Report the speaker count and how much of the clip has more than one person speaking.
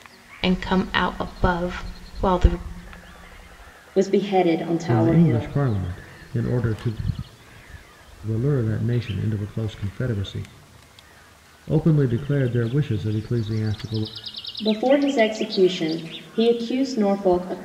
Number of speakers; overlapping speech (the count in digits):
3, about 4%